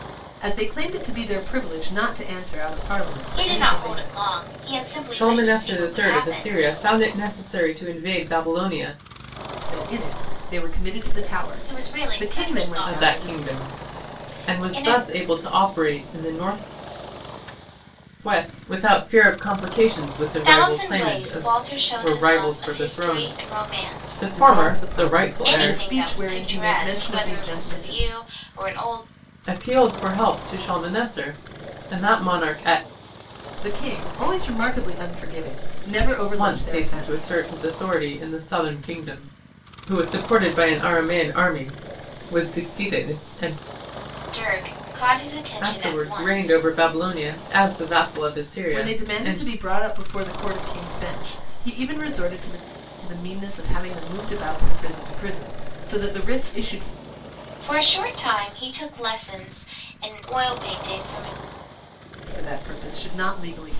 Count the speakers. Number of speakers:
3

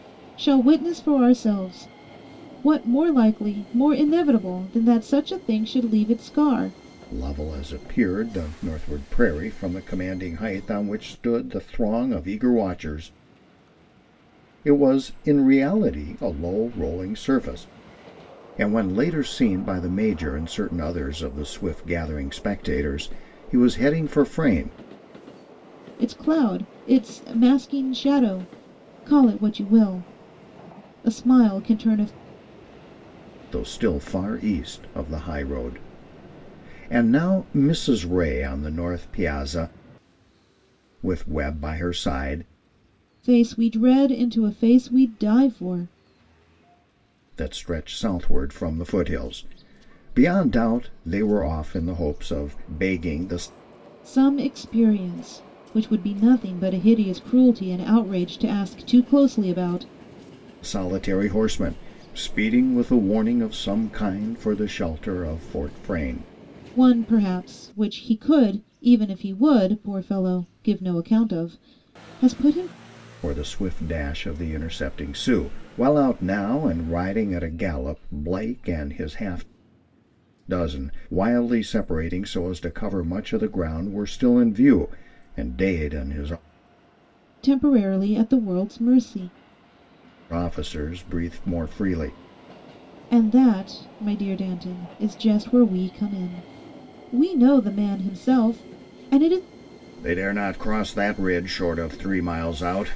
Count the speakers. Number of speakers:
2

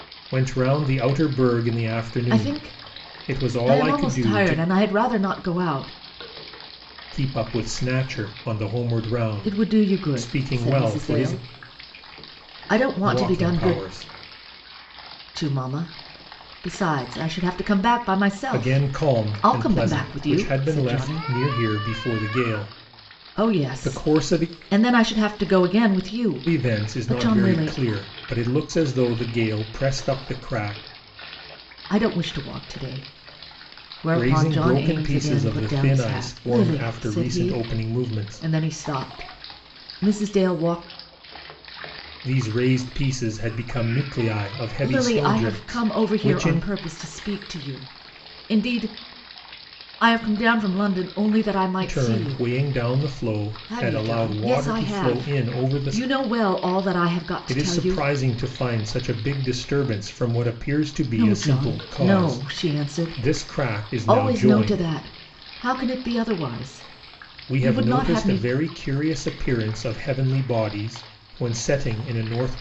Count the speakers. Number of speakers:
2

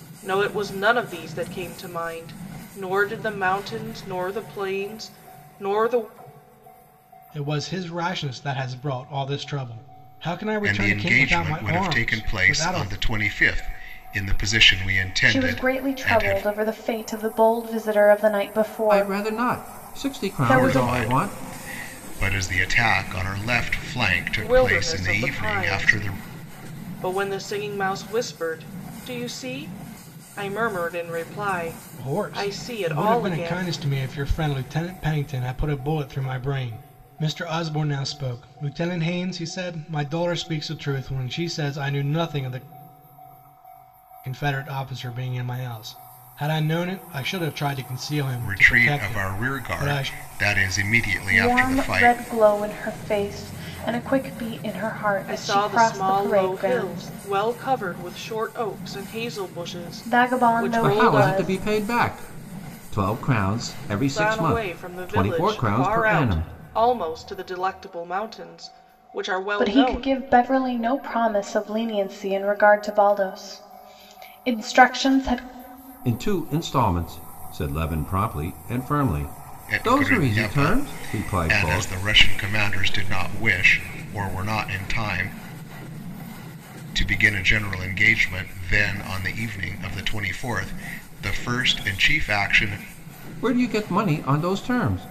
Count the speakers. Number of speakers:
5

